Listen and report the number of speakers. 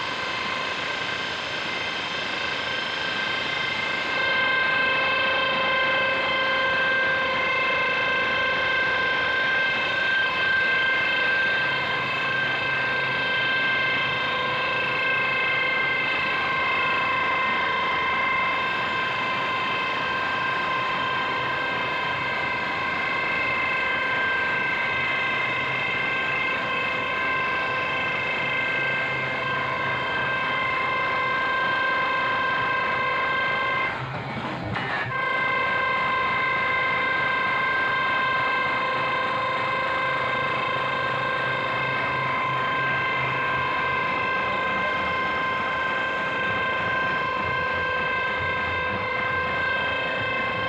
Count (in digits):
0